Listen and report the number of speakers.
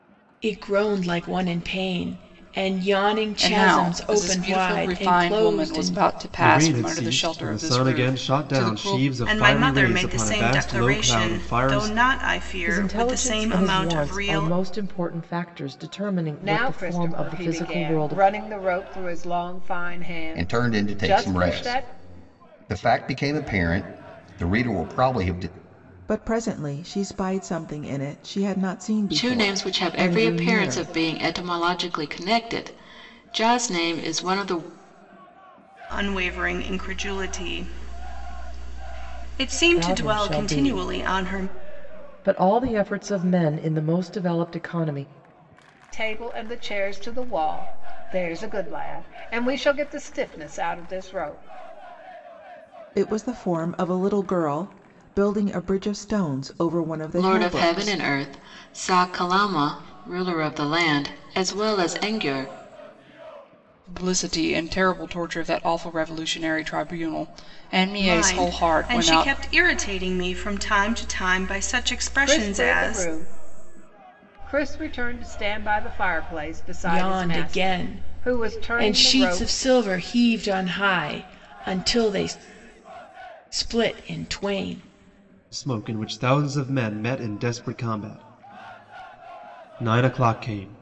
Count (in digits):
9